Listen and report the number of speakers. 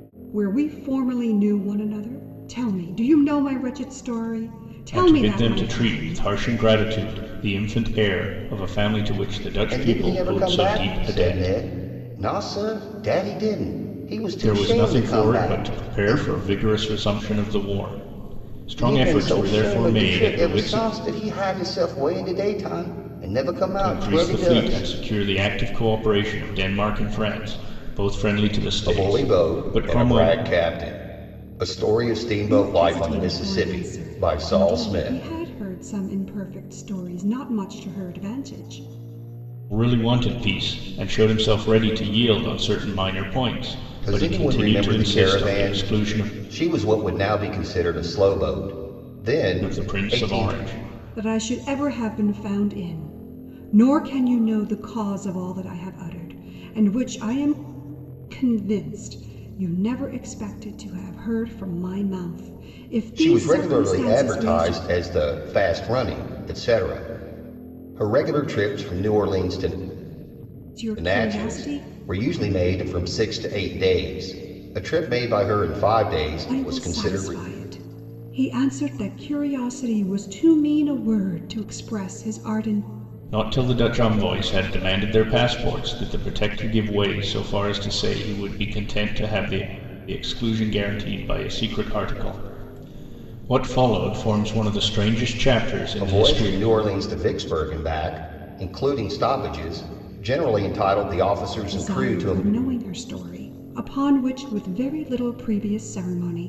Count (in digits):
3